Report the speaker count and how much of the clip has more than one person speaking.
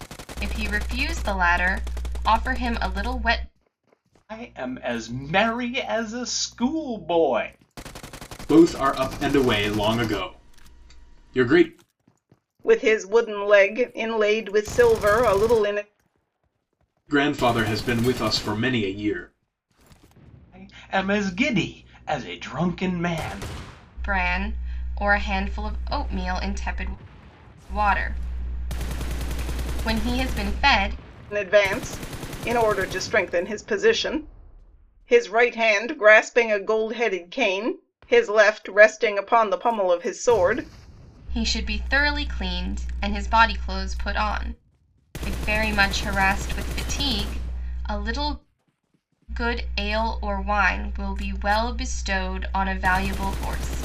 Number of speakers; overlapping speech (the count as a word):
four, no overlap